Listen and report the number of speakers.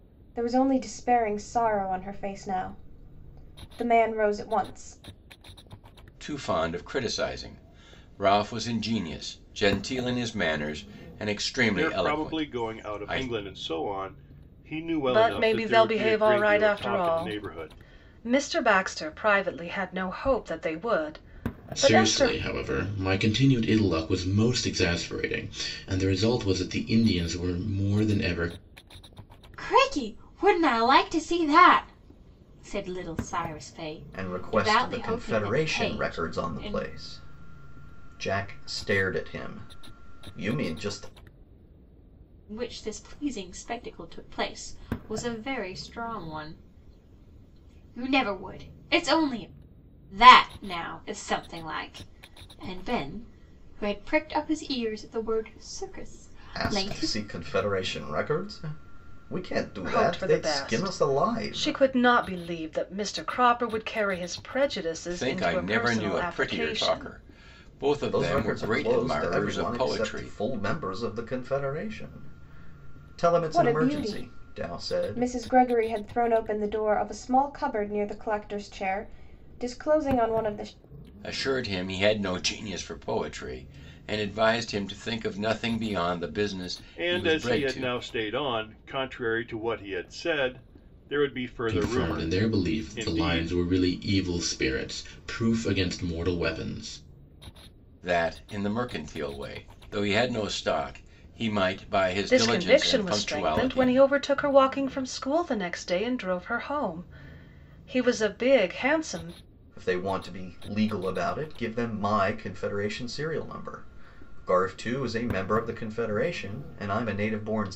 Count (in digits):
7